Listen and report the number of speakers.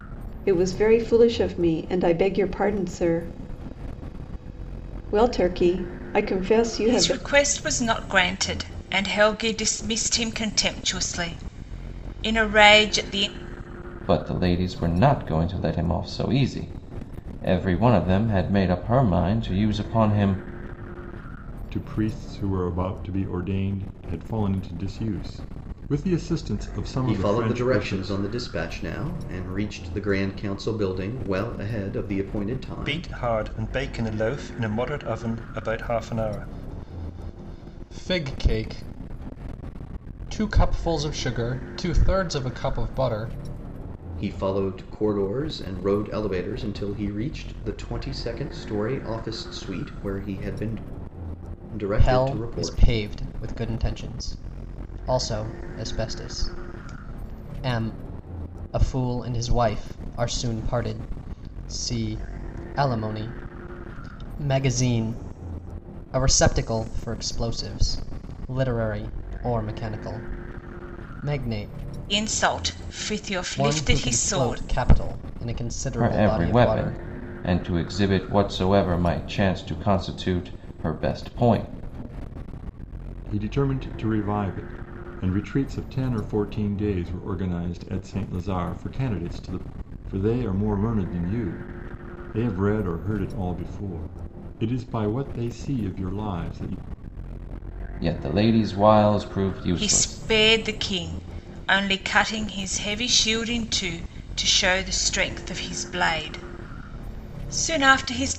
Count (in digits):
6